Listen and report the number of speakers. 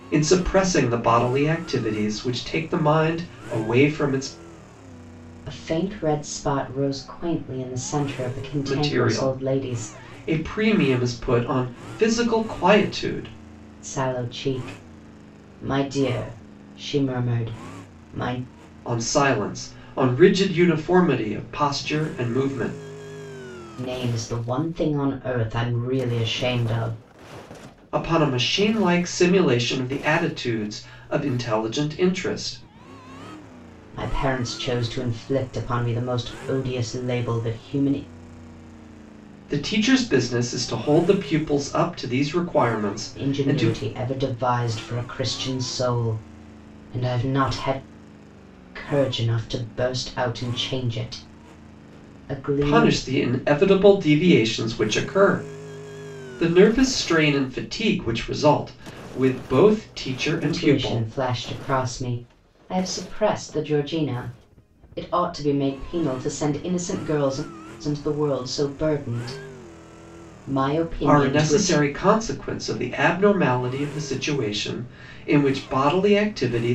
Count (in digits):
2